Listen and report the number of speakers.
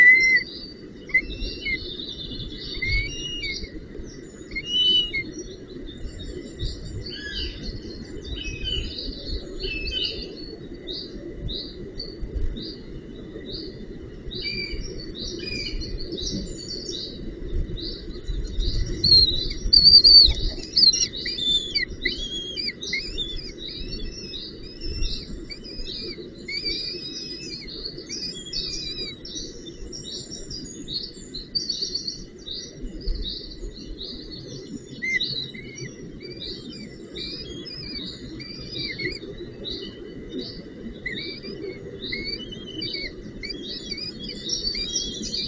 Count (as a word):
zero